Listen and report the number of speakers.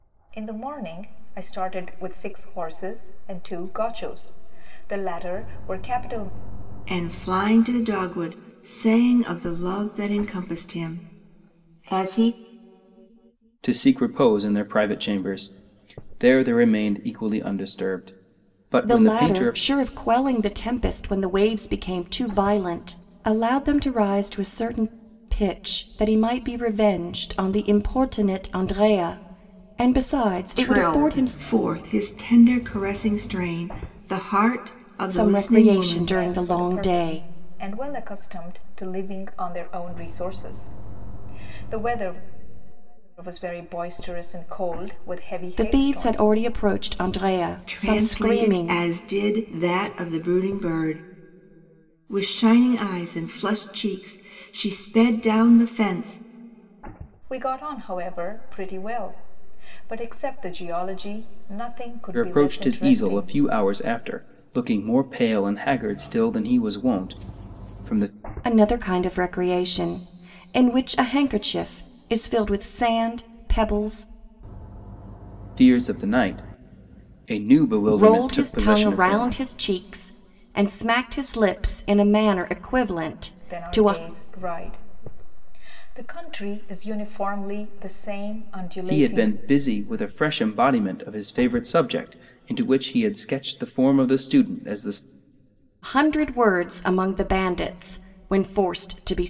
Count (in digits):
4